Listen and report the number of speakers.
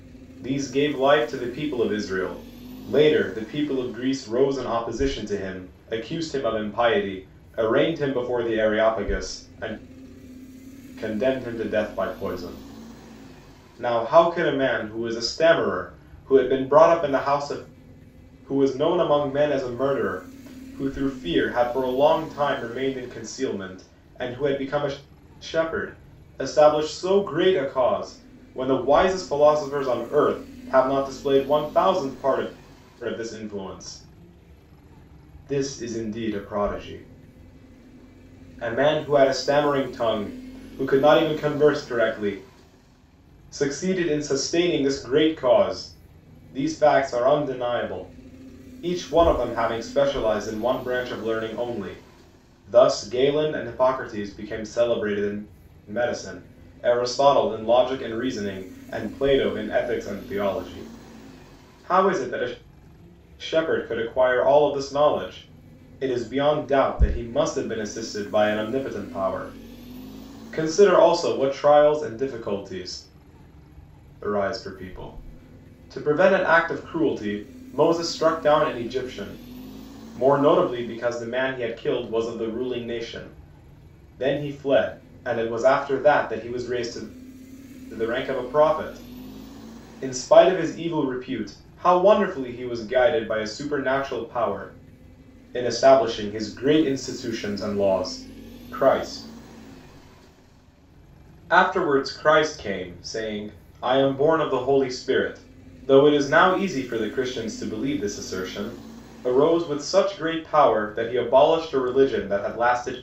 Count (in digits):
1